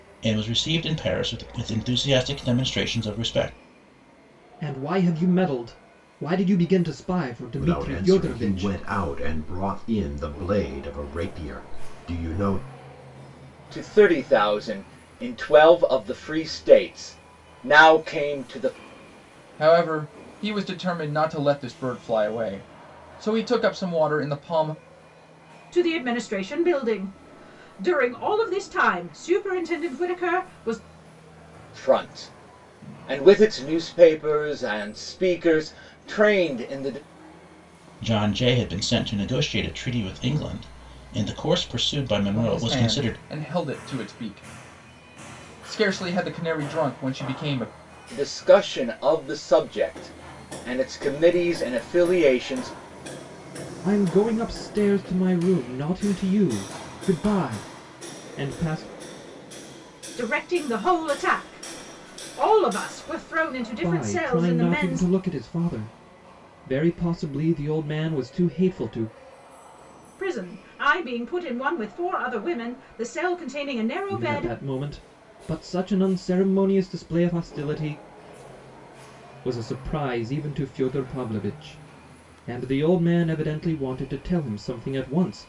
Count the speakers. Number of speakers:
6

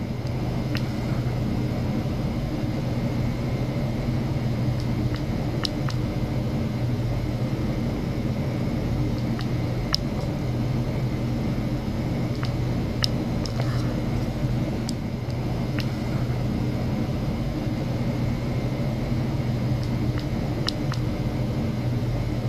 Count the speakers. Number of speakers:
0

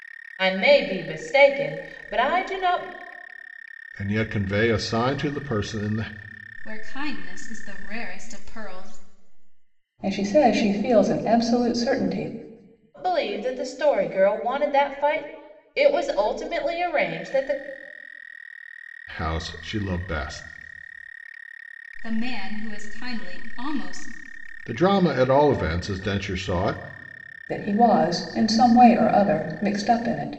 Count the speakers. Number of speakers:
4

